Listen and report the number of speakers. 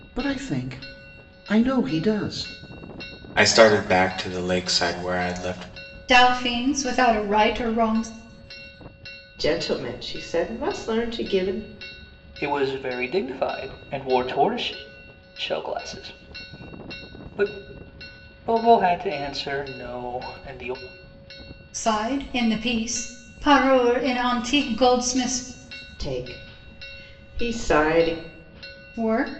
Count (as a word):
five